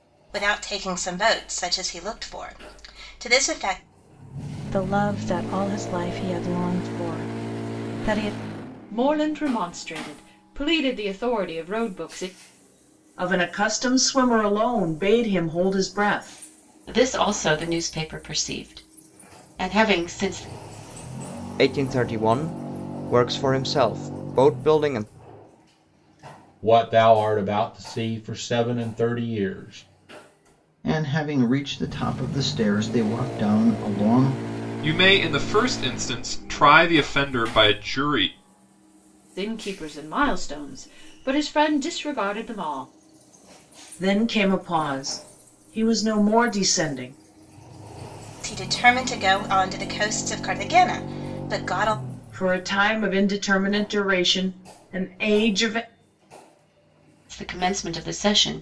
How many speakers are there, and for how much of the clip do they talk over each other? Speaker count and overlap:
9, no overlap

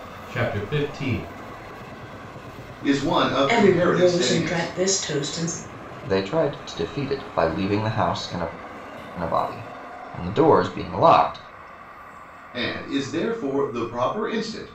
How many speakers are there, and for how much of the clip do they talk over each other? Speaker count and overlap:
4, about 8%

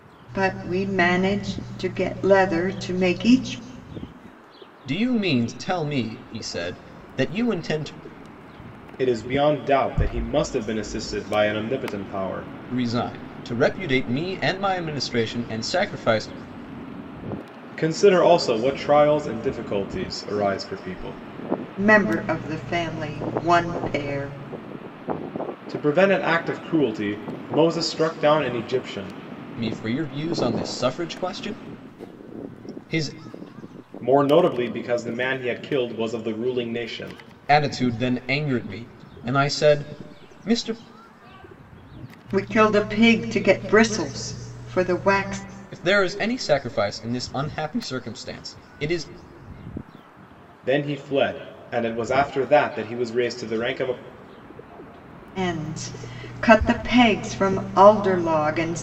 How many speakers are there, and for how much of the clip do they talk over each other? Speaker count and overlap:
3, no overlap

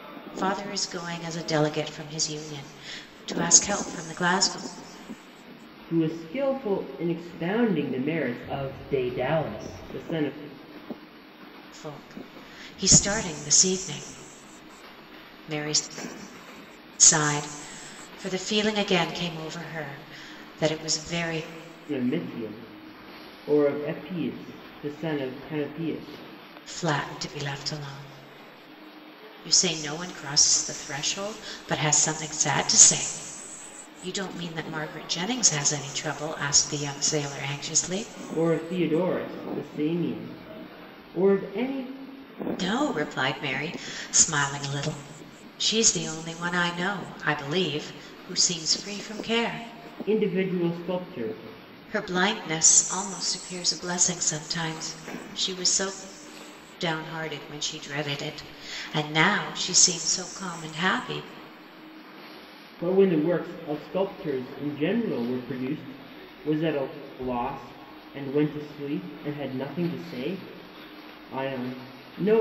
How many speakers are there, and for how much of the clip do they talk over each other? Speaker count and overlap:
2, no overlap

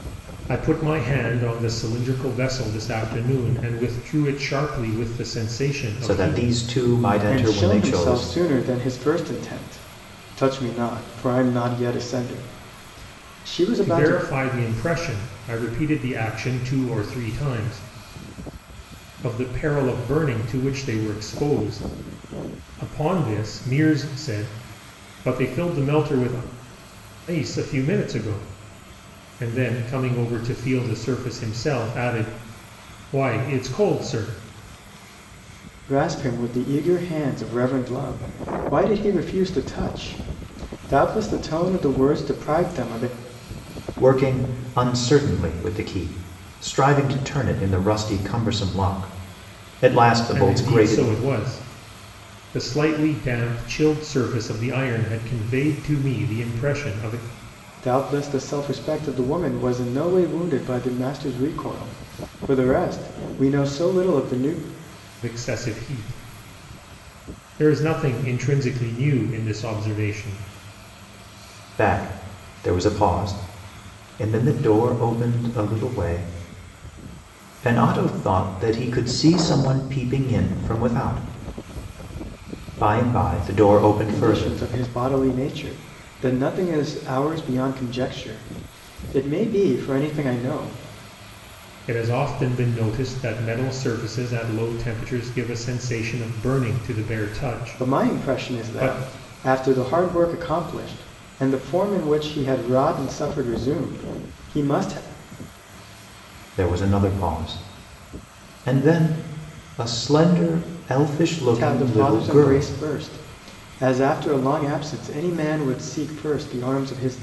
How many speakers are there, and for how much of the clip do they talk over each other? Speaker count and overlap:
3, about 5%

